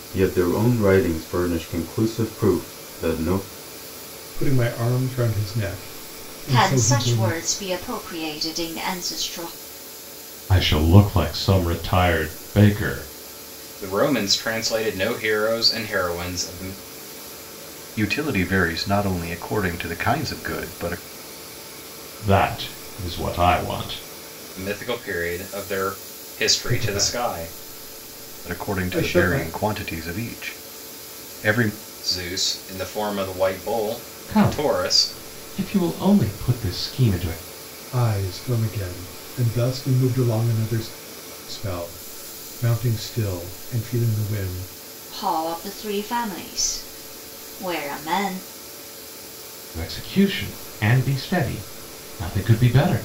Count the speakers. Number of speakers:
6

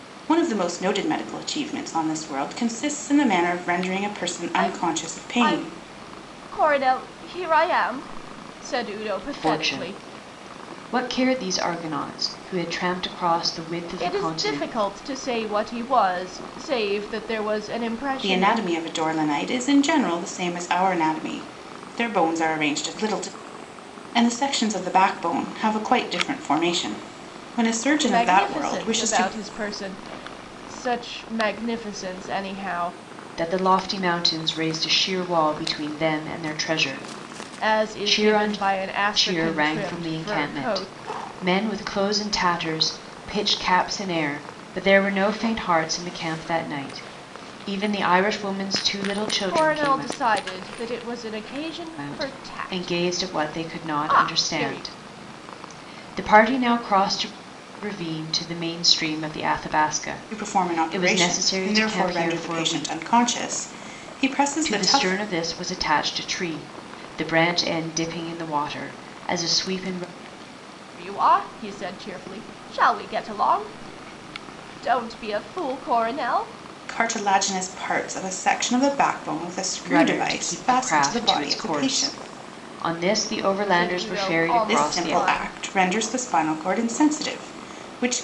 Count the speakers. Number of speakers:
3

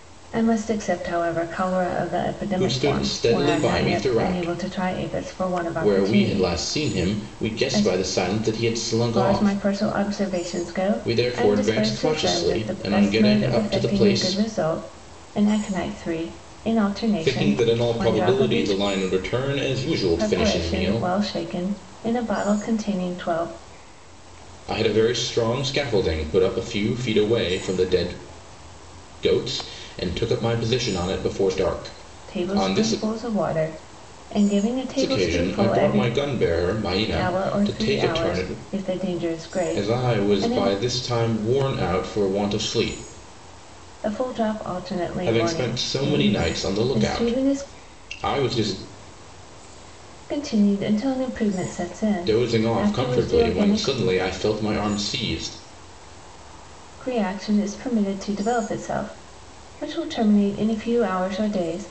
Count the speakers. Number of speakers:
2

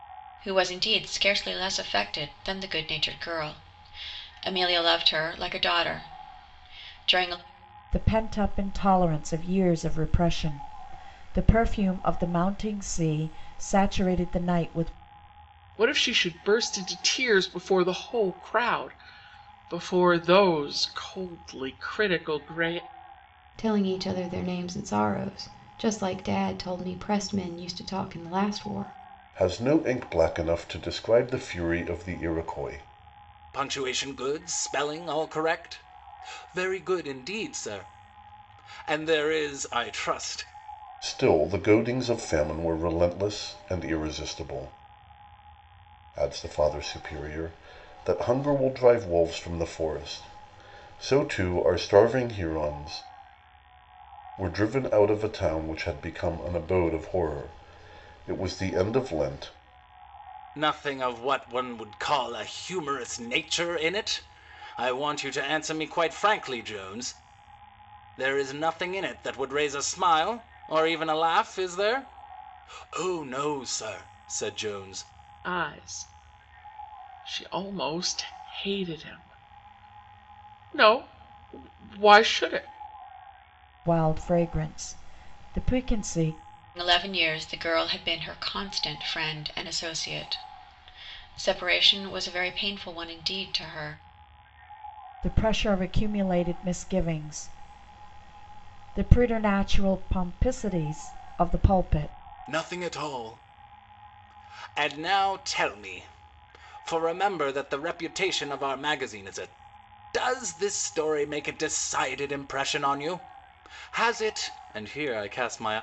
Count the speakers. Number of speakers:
6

